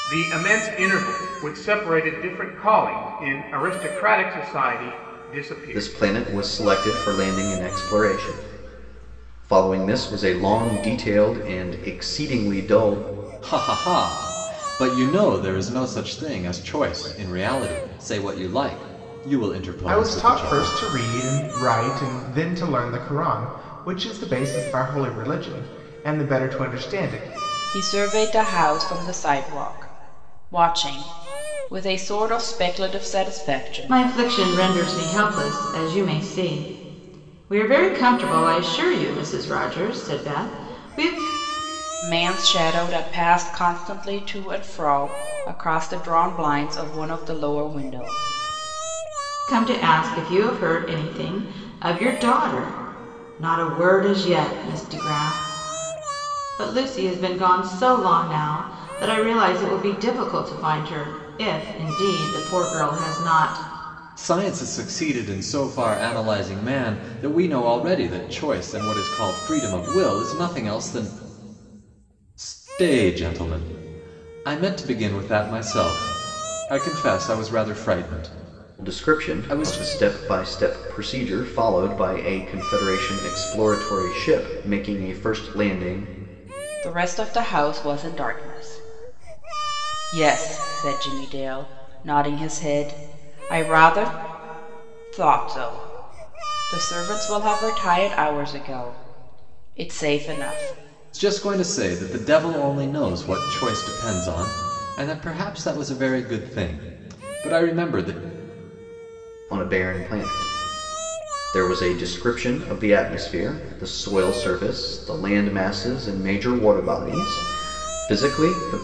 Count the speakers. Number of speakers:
6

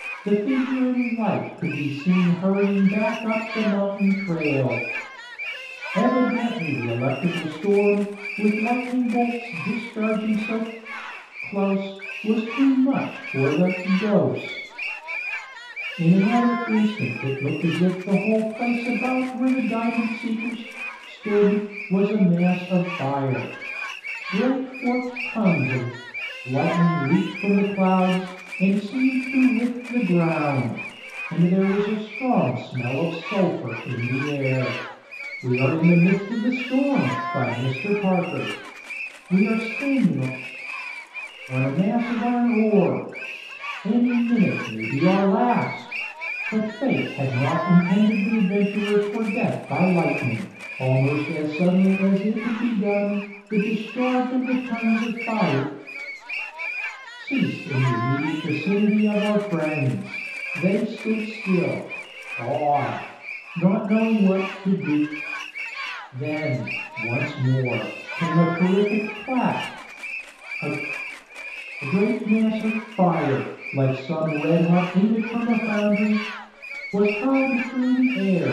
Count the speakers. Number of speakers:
1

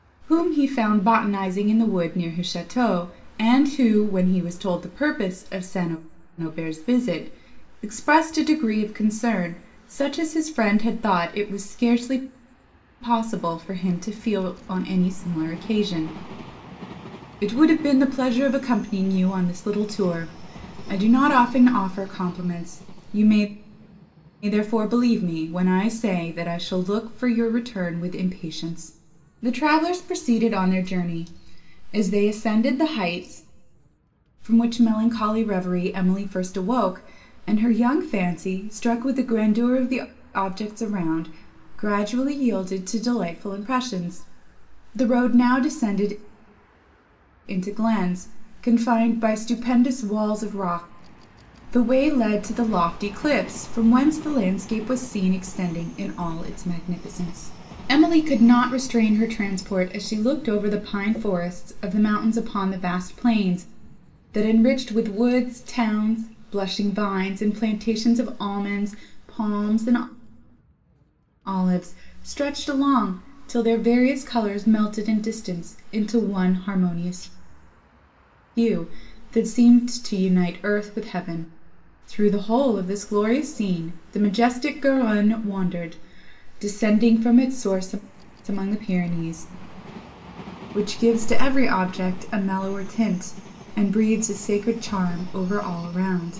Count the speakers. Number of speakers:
1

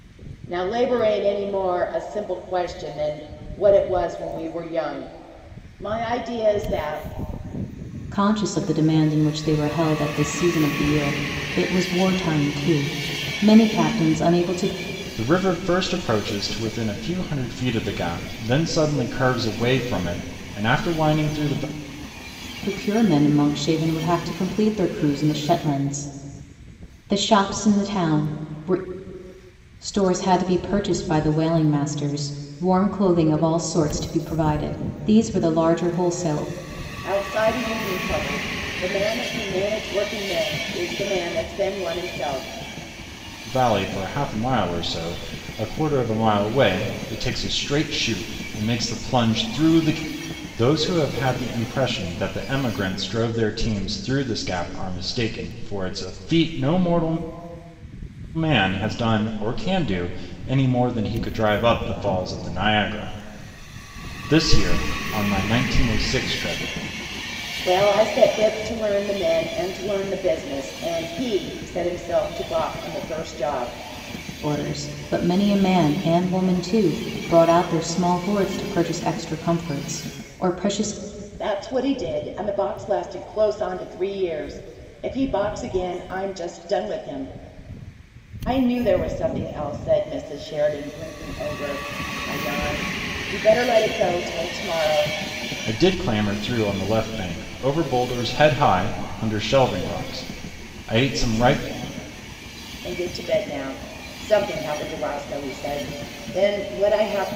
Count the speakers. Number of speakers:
3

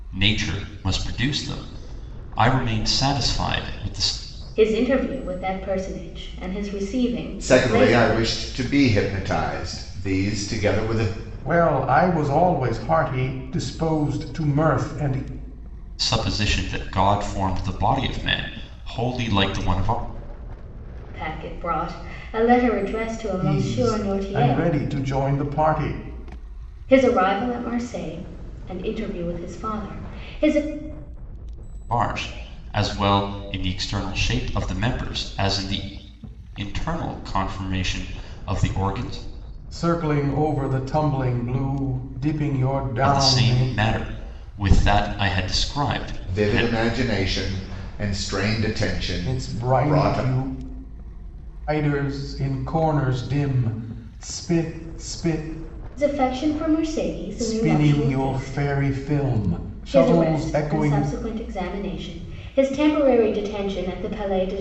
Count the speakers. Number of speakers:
4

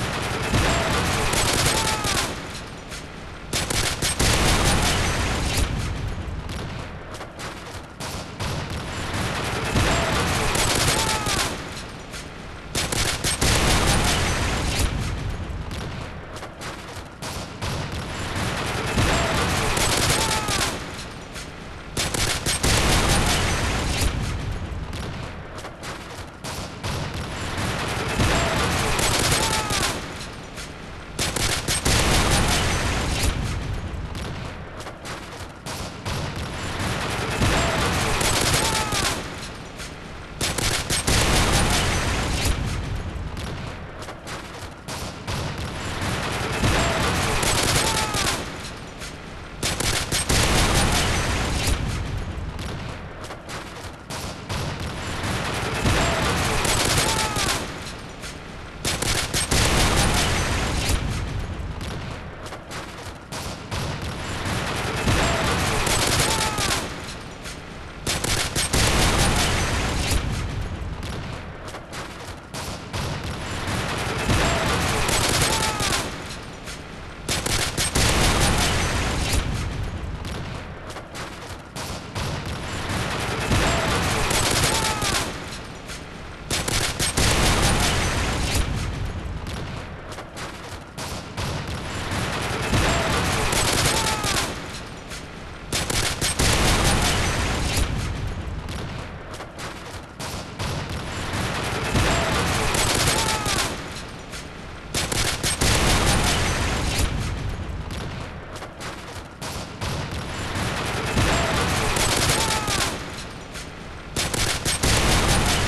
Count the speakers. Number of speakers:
0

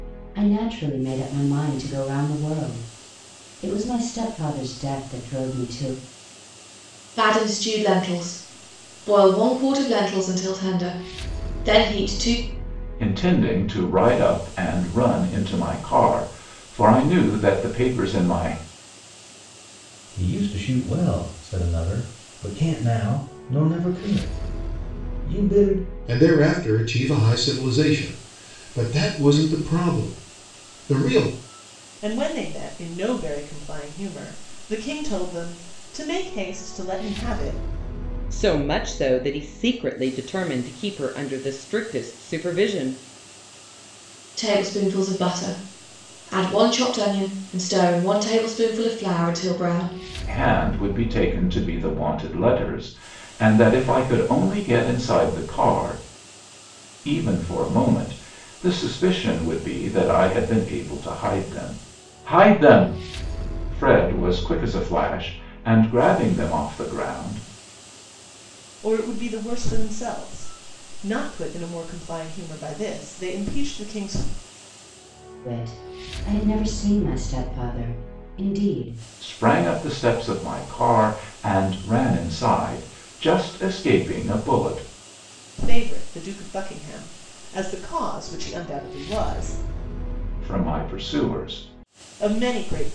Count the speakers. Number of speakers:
7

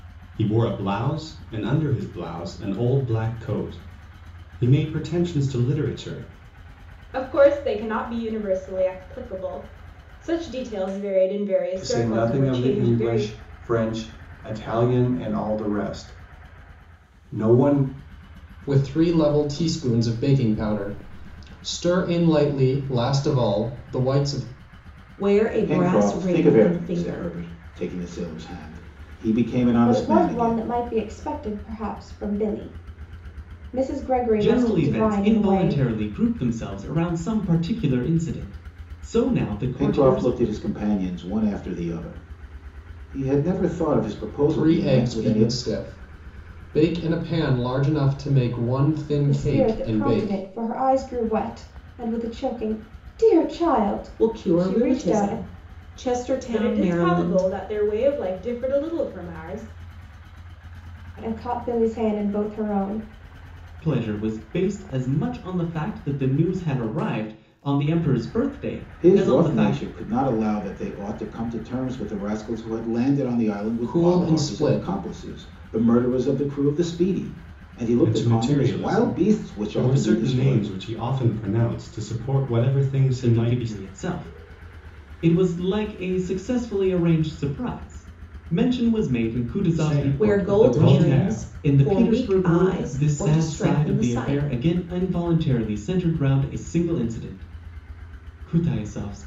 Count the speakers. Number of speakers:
8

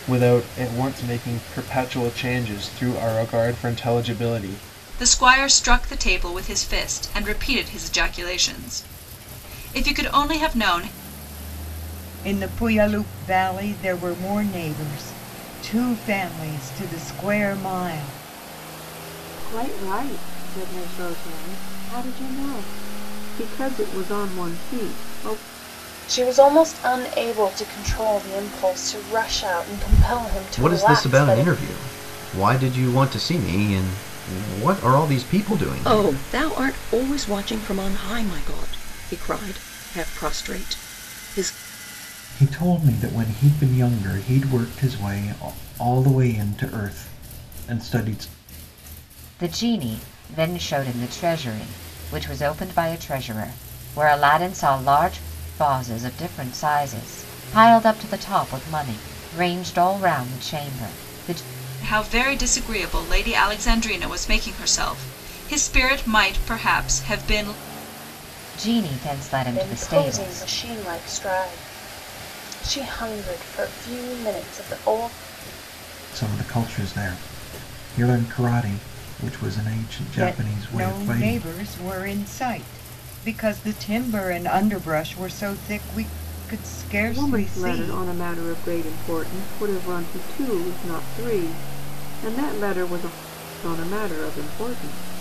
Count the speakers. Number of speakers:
9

